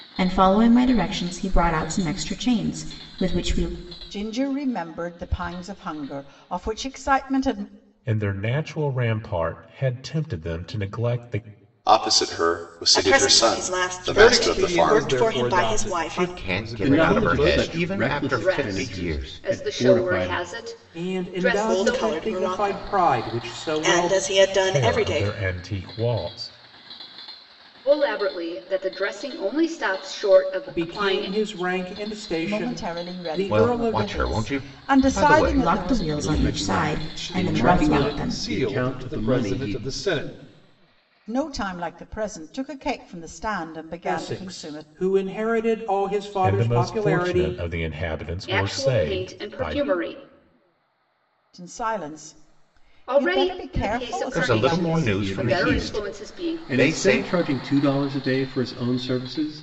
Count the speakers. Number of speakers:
10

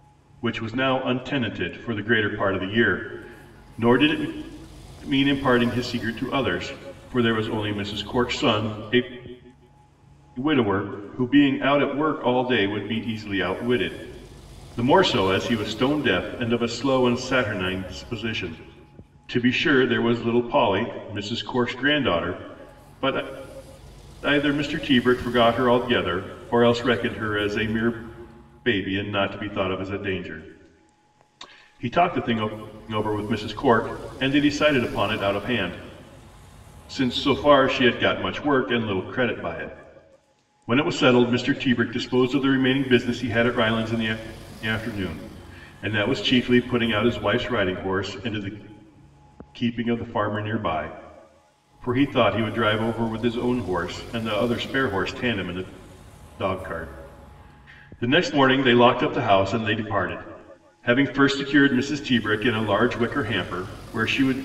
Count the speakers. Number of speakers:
1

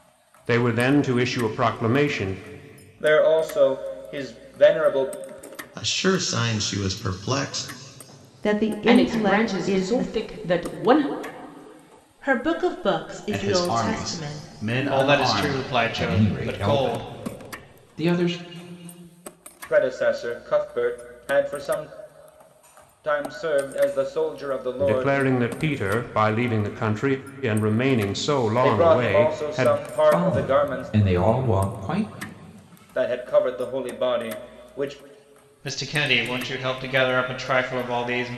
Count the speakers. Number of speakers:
9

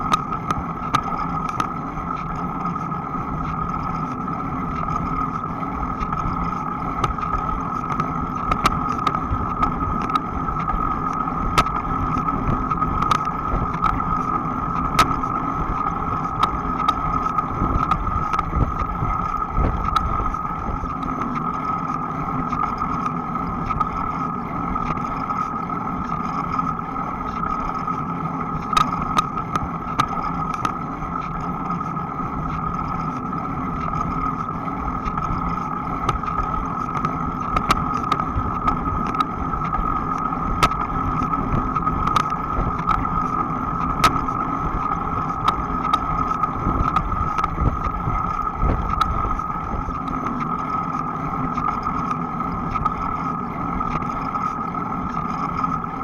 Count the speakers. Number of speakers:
0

